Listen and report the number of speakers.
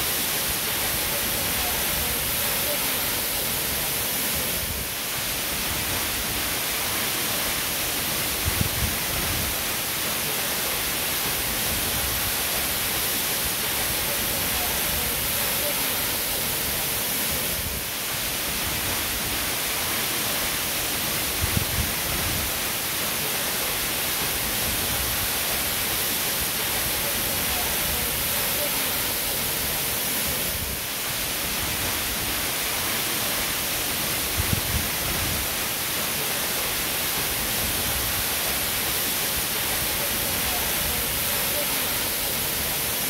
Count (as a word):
zero